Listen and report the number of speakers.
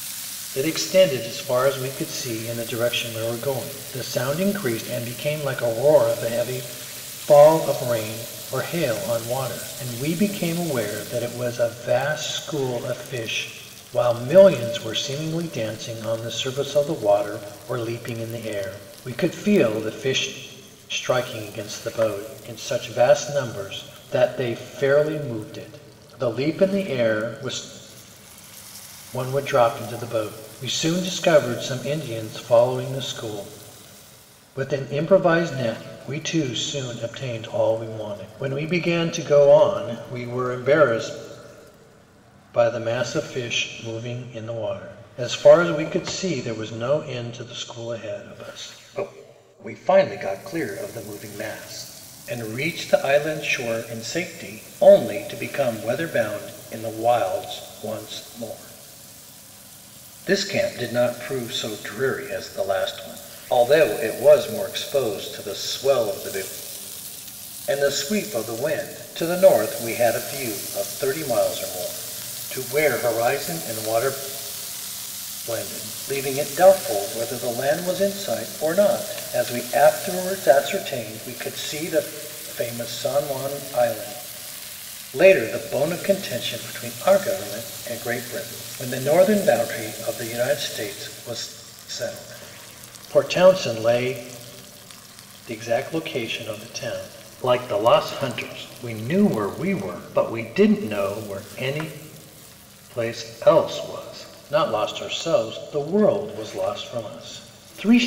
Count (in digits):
1